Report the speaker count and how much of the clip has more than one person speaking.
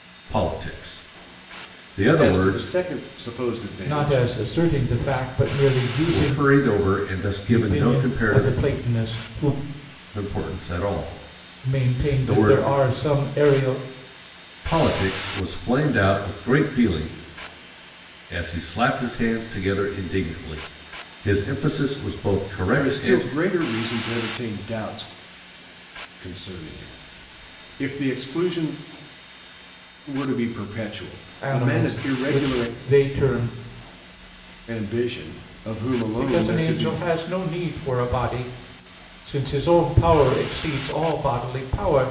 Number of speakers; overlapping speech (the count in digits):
3, about 15%